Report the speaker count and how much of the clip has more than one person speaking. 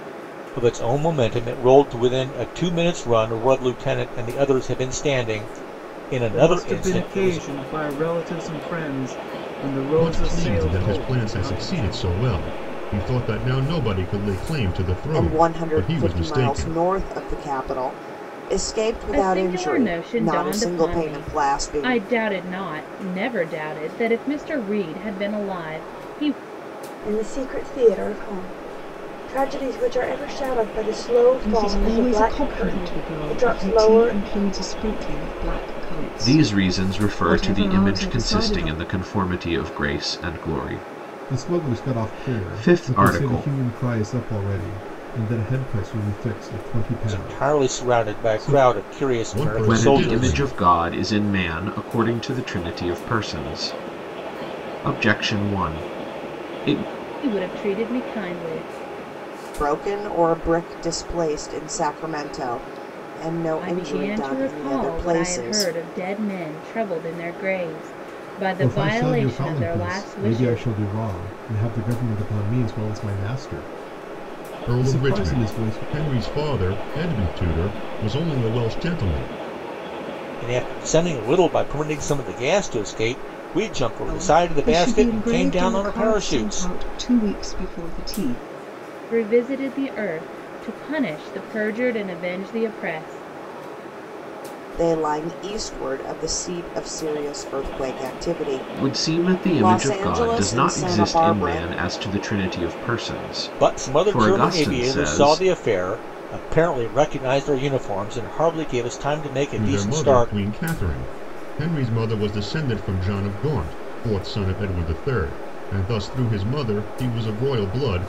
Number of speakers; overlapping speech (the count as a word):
nine, about 27%